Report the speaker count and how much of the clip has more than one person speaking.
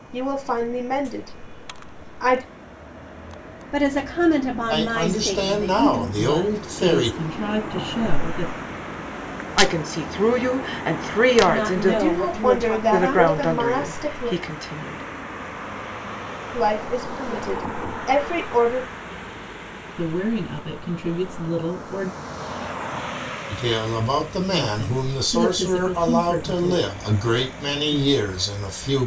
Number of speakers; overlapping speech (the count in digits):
5, about 26%